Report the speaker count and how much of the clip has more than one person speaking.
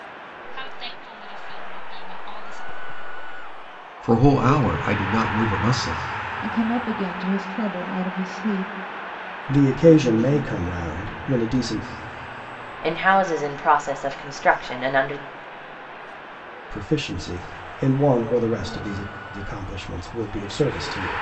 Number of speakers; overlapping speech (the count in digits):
5, no overlap